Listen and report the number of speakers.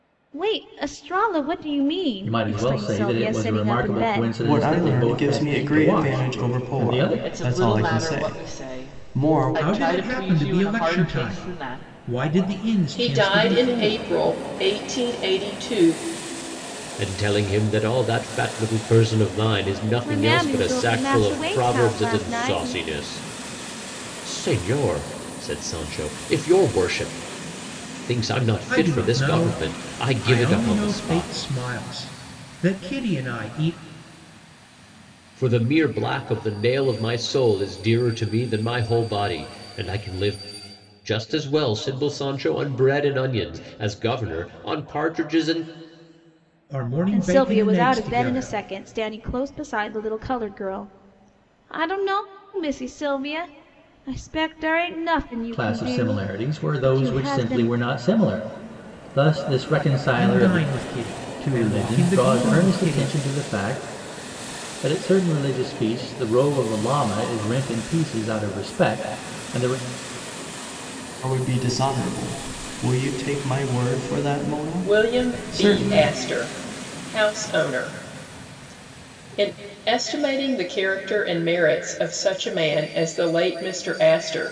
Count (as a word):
seven